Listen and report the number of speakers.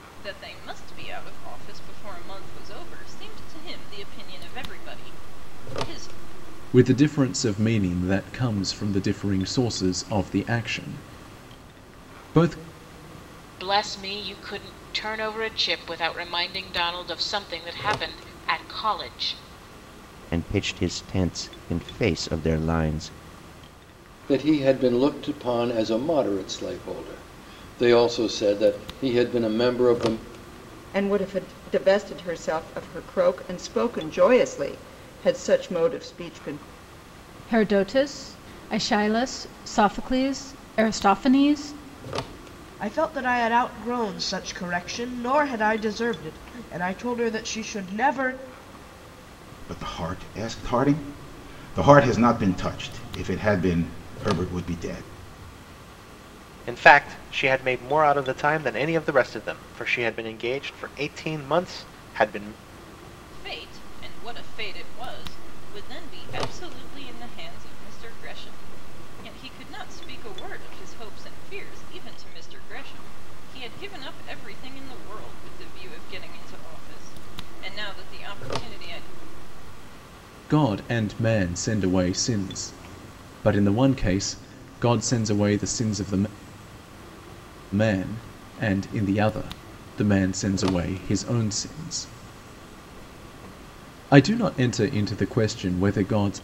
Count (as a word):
ten